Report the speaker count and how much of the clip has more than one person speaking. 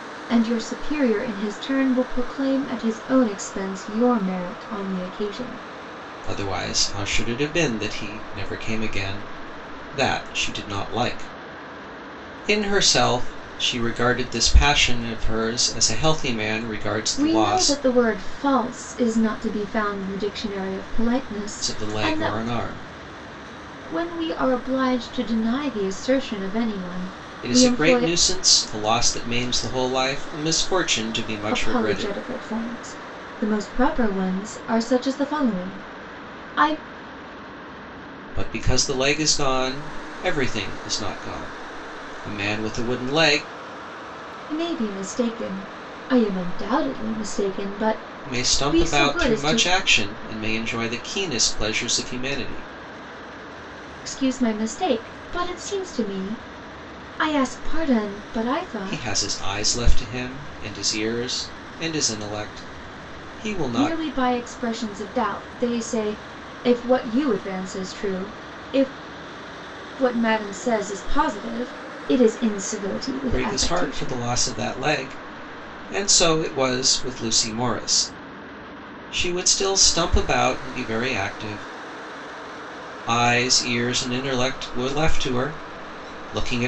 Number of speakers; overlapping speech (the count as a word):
two, about 7%